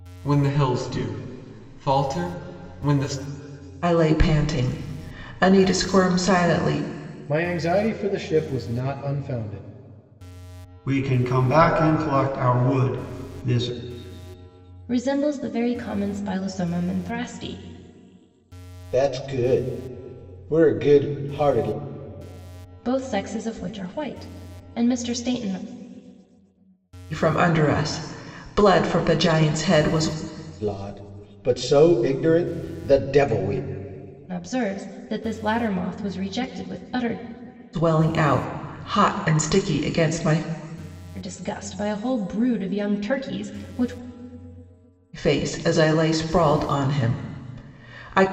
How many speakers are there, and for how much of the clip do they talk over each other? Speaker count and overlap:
6, no overlap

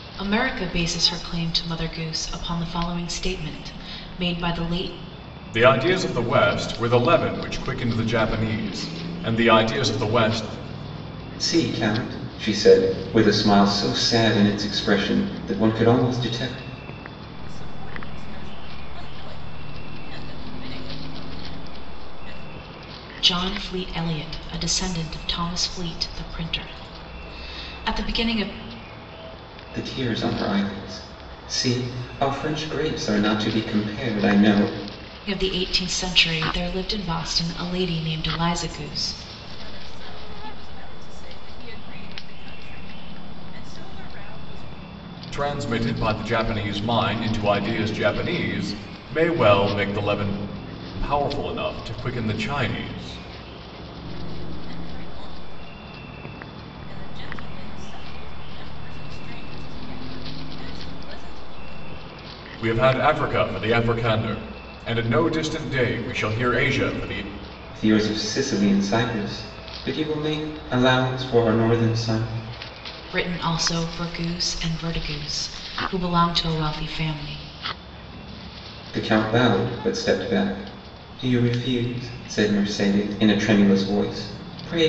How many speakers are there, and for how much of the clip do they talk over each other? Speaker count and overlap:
4, no overlap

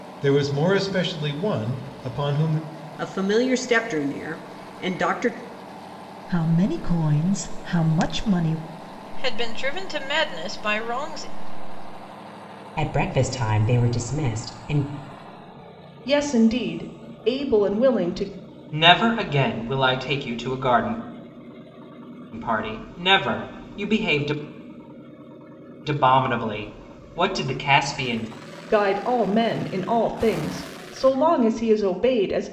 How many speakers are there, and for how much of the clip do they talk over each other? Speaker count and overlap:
7, no overlap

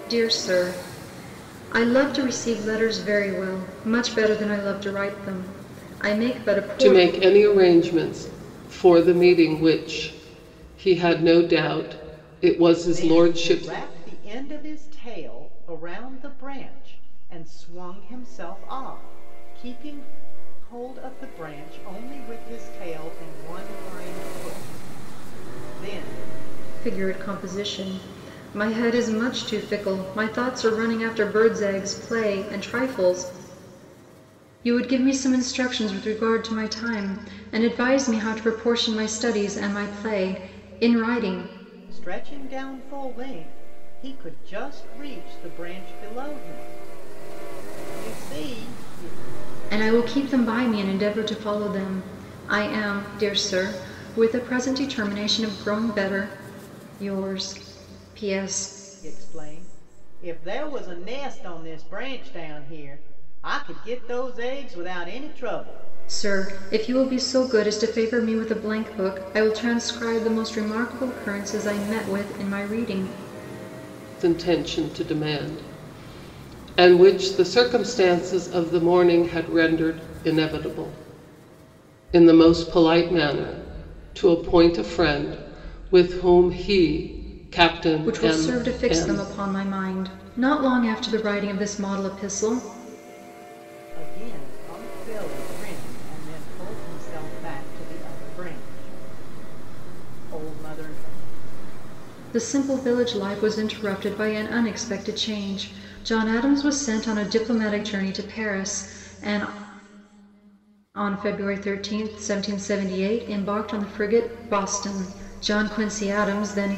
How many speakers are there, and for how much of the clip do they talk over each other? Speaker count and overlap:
3, about 2%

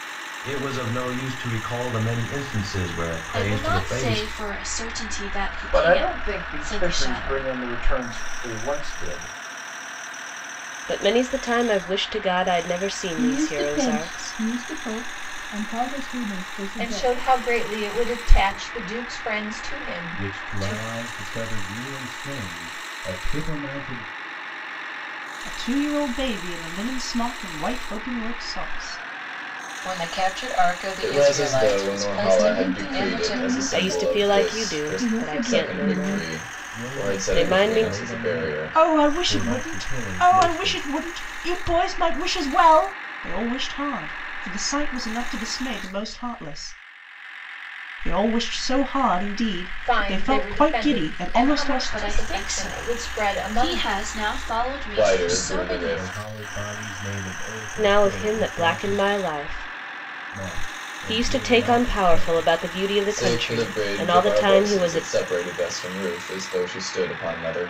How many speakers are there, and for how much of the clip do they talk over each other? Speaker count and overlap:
10, about 38%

